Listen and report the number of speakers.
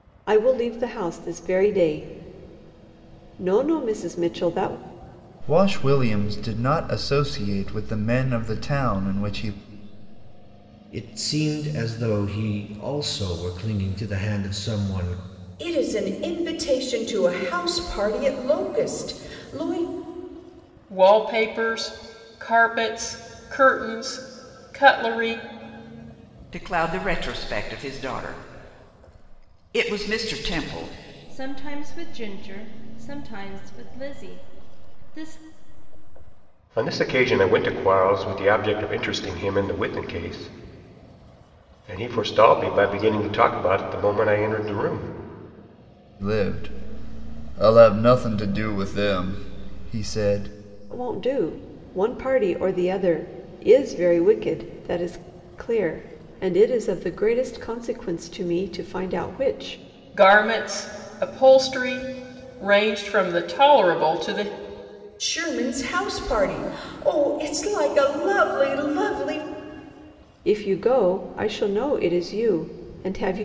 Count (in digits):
8